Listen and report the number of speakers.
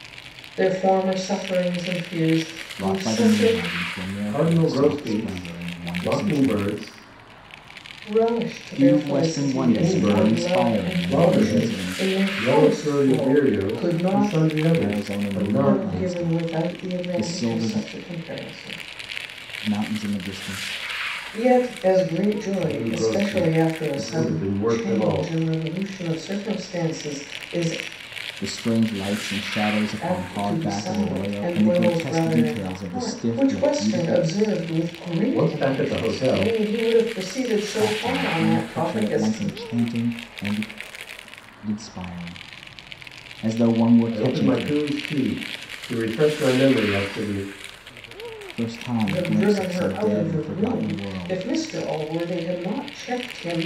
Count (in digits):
3